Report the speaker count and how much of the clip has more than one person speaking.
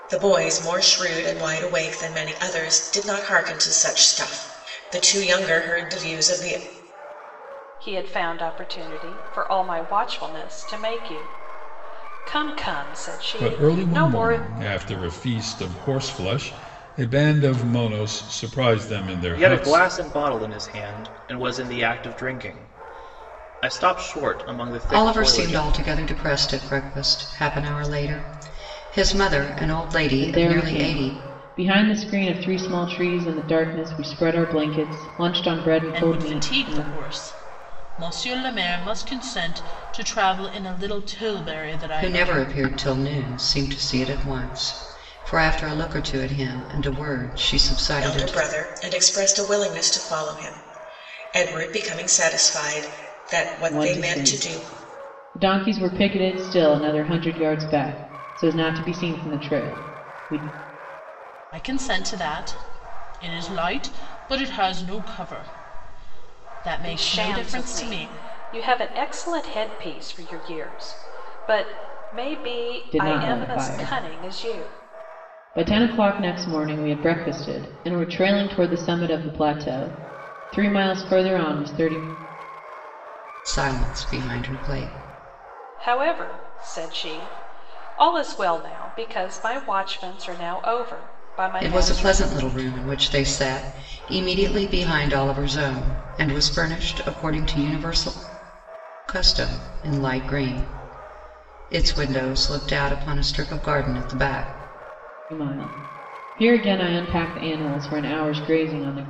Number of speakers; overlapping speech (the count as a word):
seven, about 9%